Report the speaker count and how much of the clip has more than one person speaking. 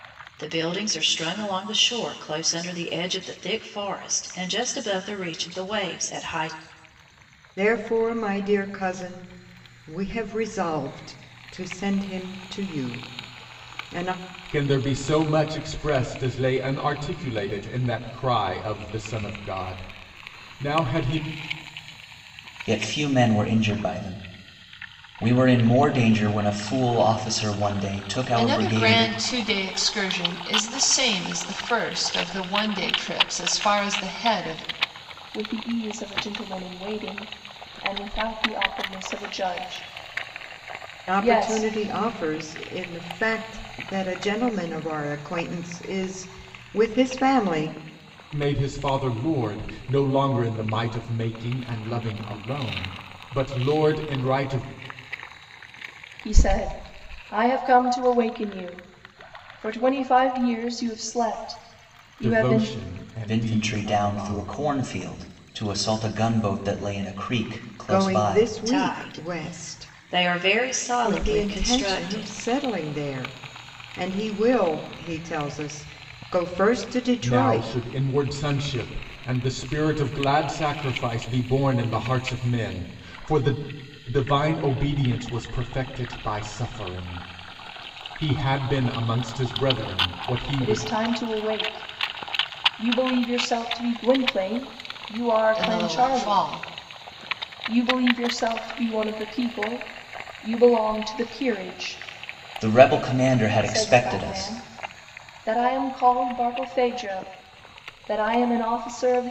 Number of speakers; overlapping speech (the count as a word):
six, about 9%